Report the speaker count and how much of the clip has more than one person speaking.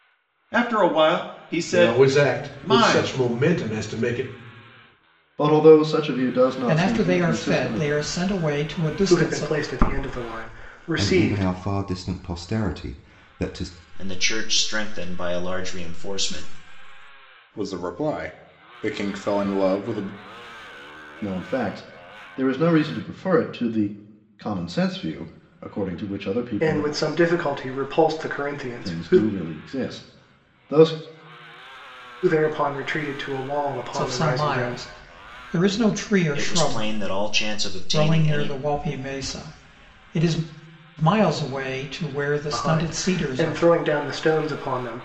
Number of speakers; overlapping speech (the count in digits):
8, about 18%